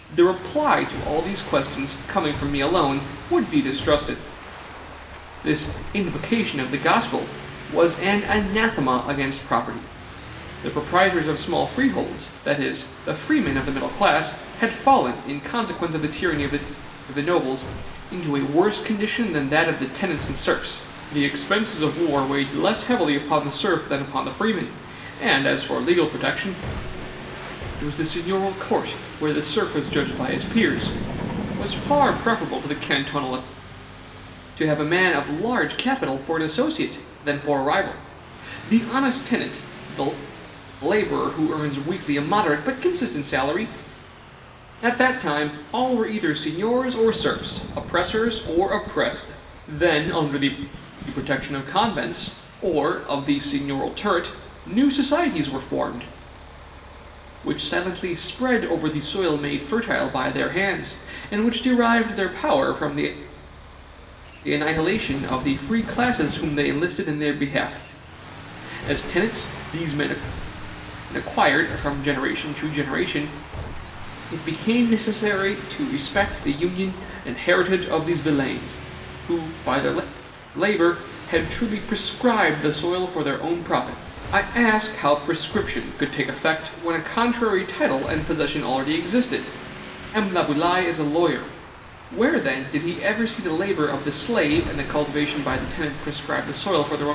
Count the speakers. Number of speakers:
1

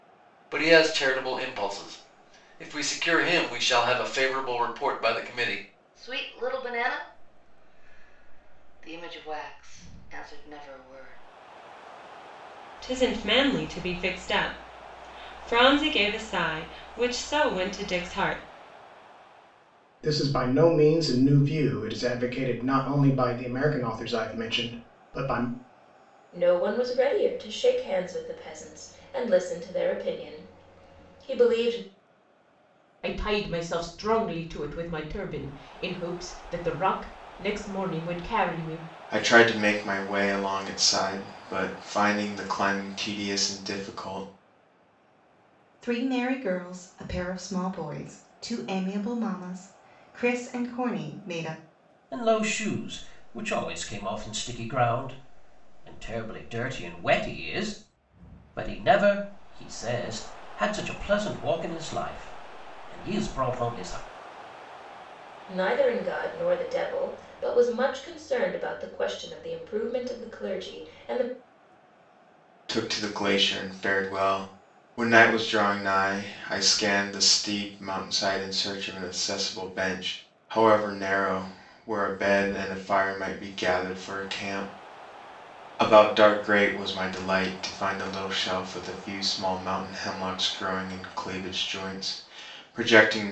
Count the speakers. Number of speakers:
9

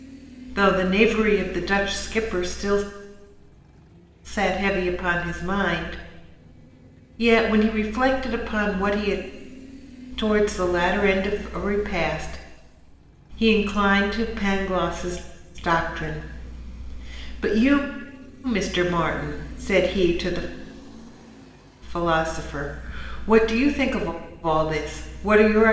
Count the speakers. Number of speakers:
1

